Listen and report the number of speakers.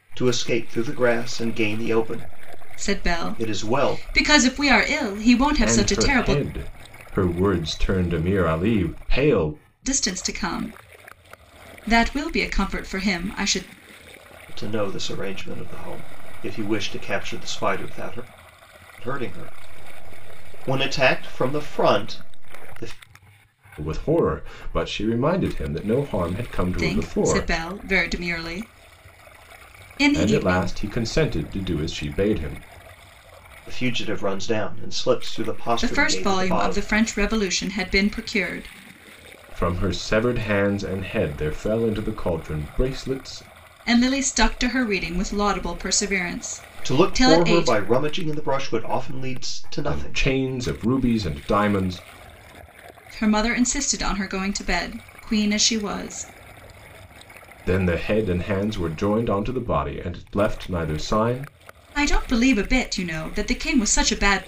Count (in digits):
3